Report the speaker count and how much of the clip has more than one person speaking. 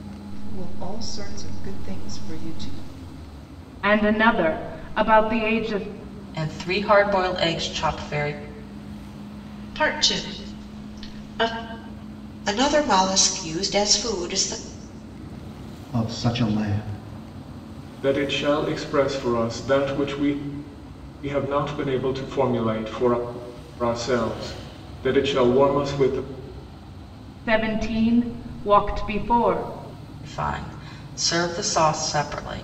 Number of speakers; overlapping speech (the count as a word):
seven, no overlap